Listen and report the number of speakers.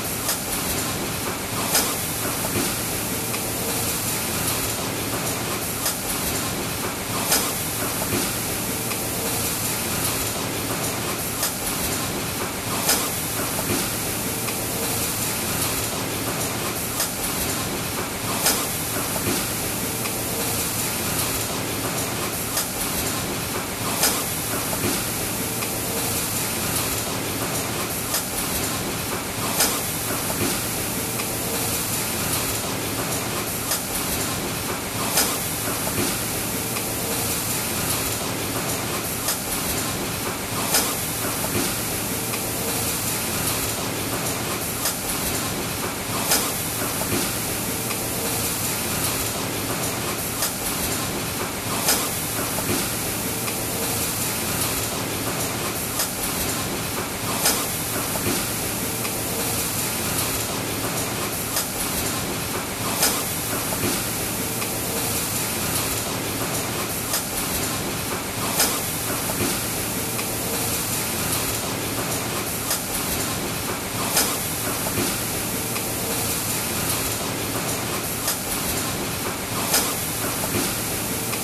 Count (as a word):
zero